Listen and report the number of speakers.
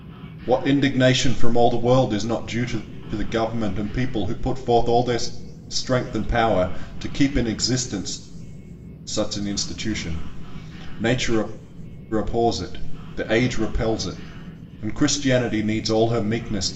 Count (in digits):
1